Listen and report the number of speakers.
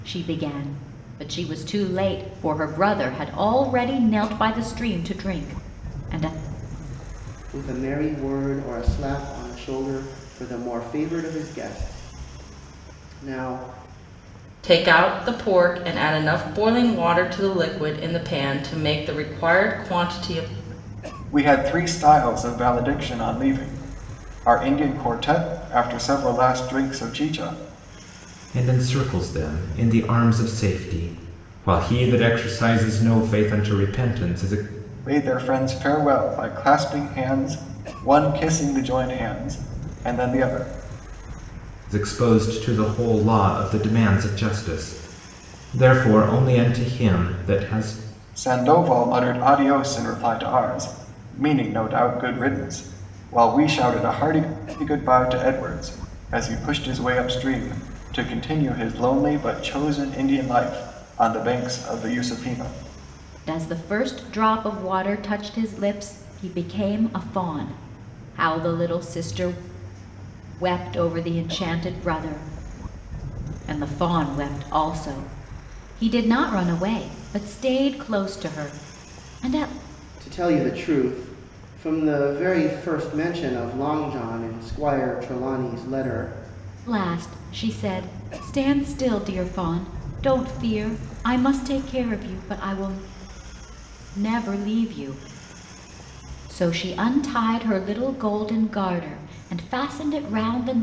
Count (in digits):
5